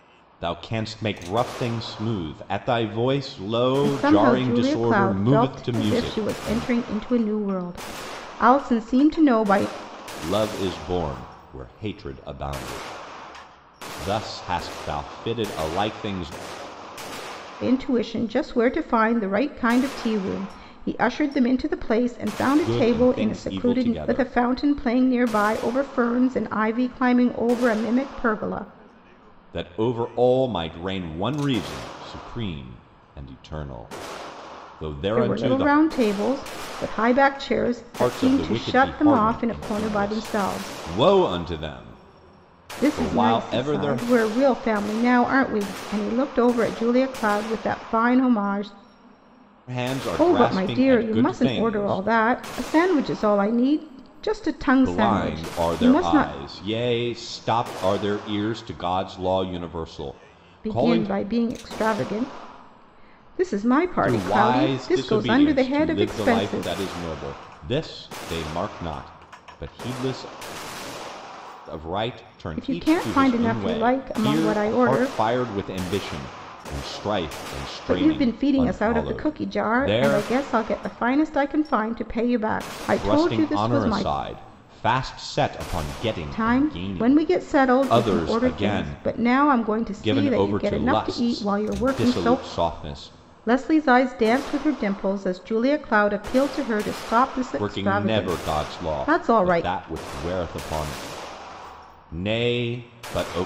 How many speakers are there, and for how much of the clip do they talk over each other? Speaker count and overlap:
two, about 29%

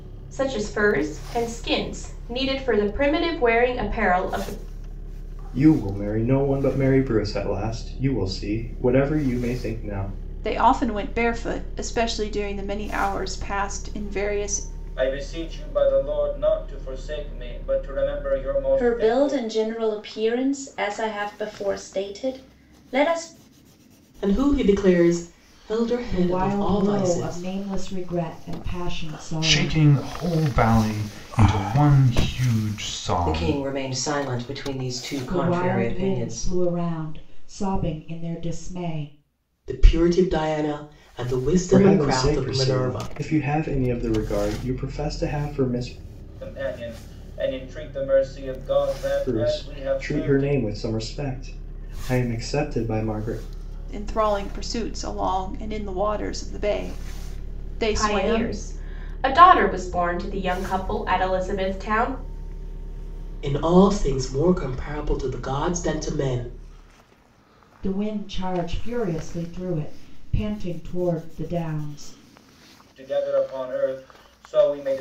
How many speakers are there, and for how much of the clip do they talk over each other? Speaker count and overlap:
nine, about 10%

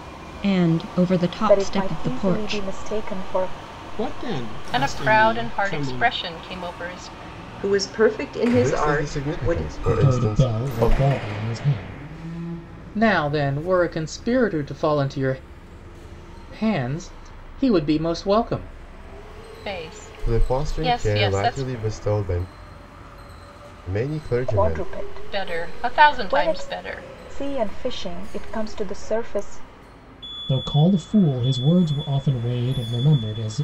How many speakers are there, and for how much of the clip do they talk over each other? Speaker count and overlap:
eight, about 25%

